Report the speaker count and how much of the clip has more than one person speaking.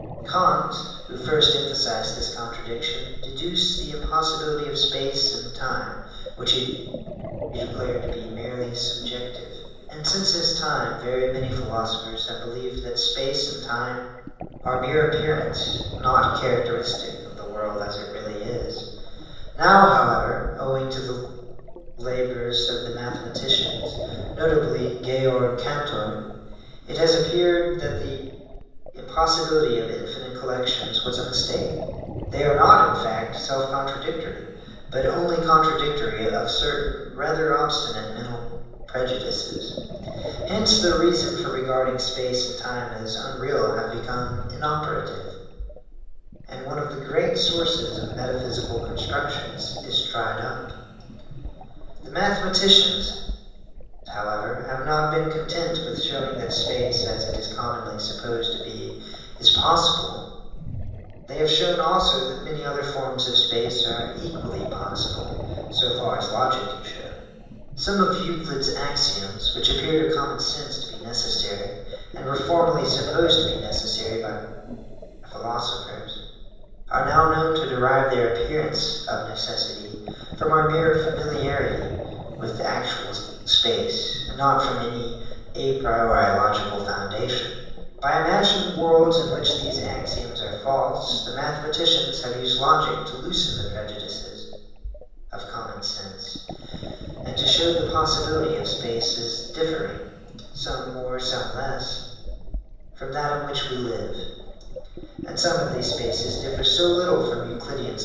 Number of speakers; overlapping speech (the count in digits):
1, no overlap